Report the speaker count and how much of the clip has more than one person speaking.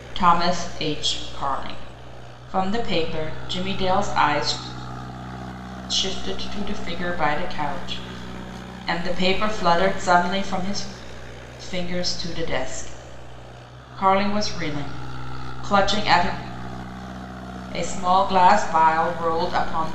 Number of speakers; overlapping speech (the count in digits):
1, no overlap